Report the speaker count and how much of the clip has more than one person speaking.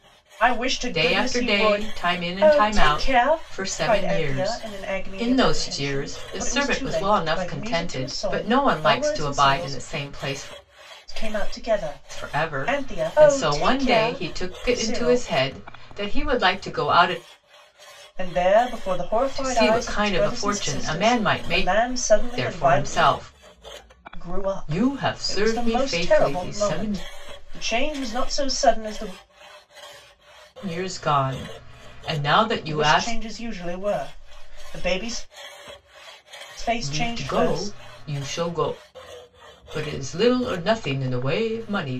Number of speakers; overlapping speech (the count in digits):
2, about 45%